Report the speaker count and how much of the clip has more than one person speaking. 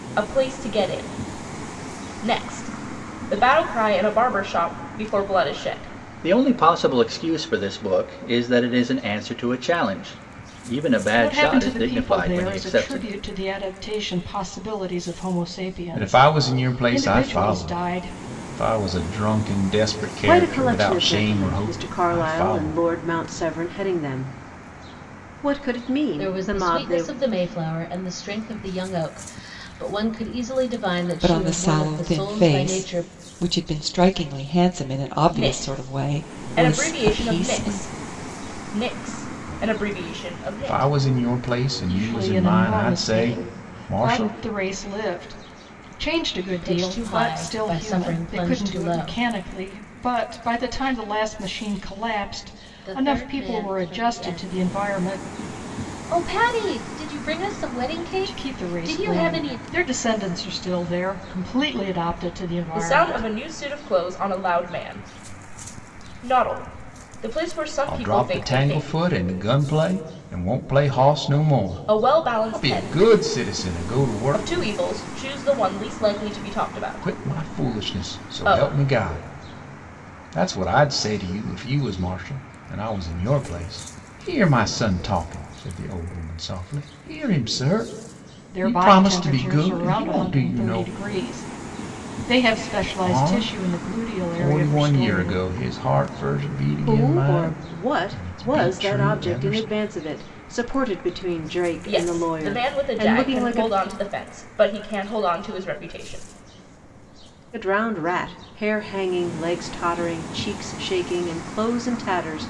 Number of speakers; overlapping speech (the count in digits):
7, about 35%